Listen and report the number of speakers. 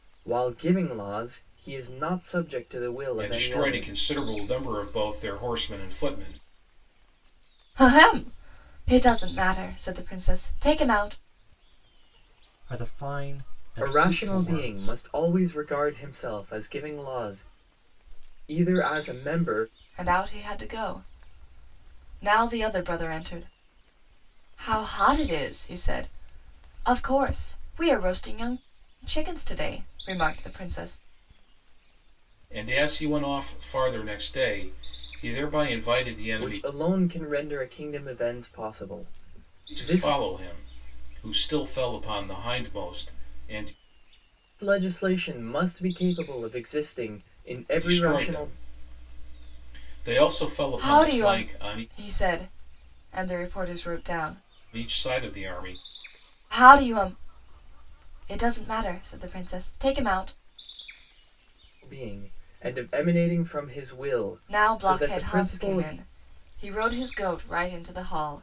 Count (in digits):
4